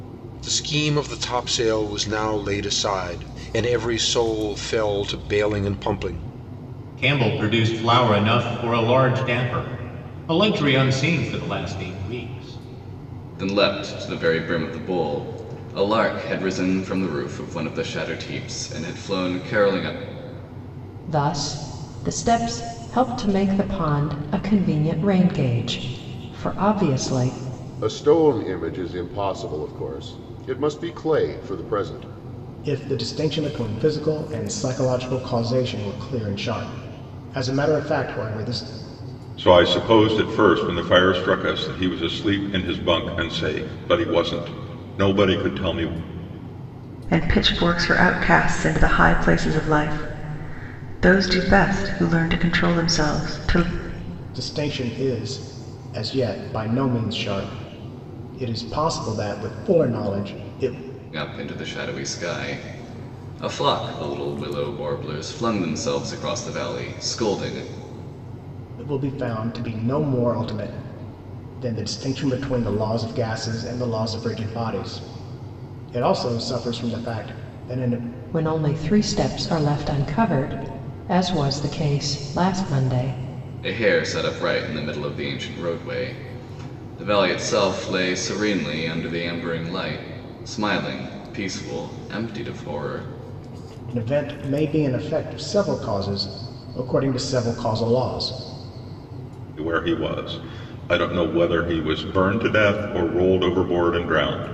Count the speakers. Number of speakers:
8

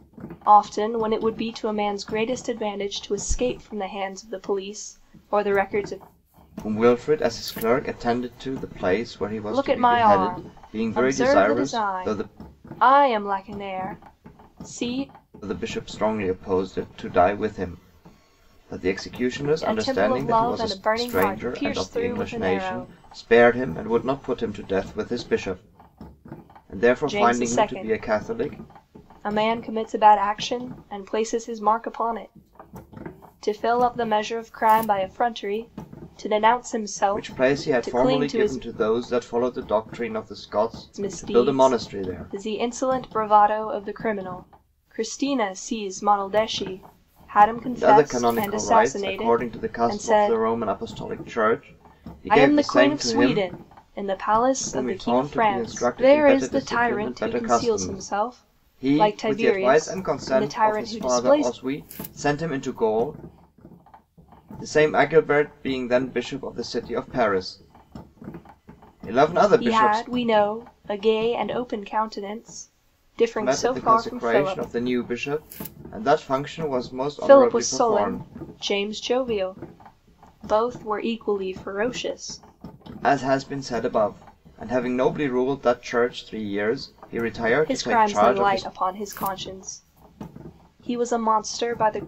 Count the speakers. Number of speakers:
2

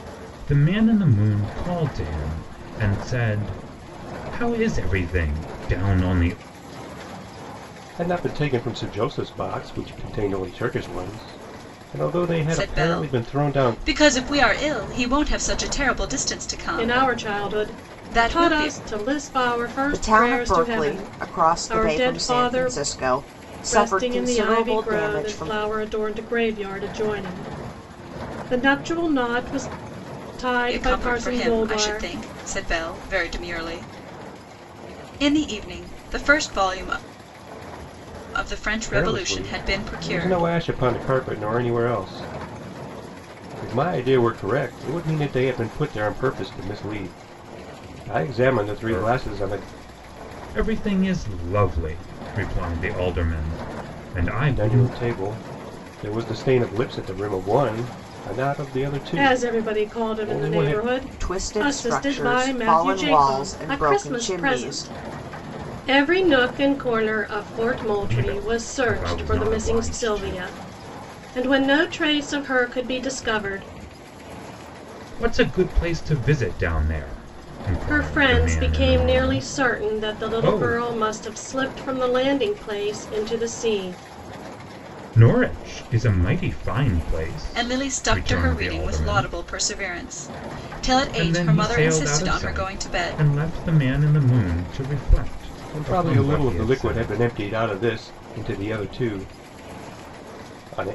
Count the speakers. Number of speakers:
5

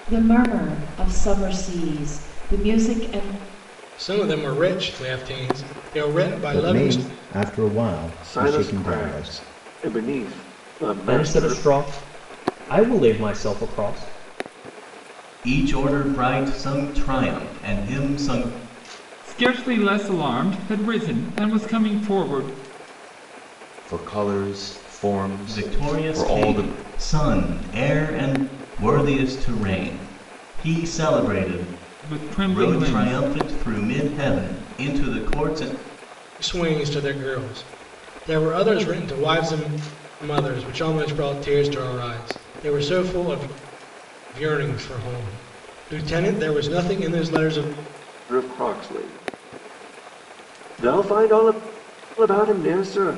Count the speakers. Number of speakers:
8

